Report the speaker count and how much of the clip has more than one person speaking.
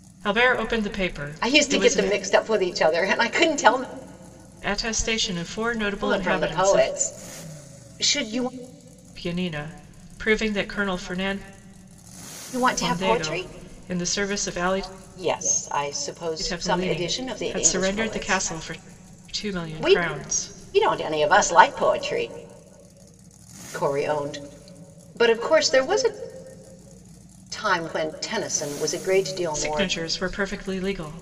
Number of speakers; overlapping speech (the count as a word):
two, about 22%